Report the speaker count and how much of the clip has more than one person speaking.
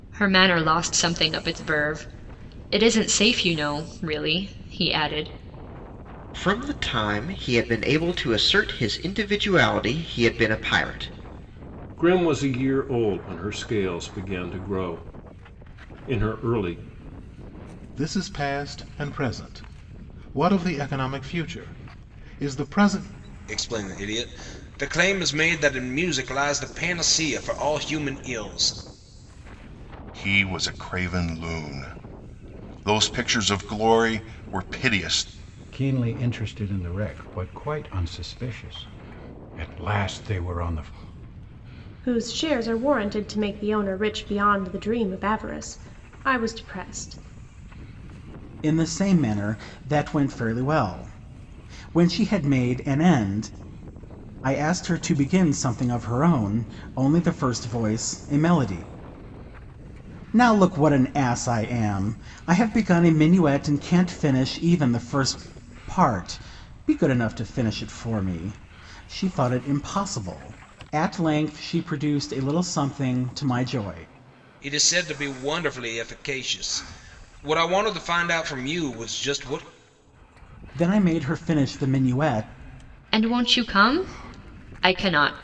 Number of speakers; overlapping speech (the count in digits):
9, no overlap